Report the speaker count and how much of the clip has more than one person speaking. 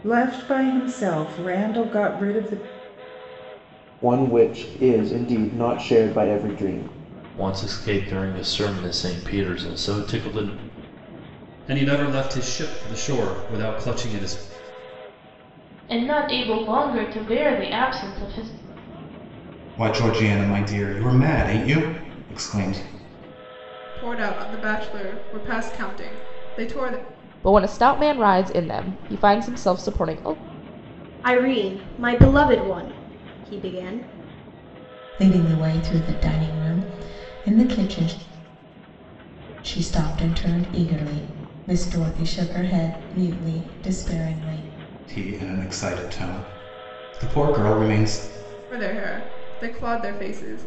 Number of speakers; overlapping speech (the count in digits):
10, no overlap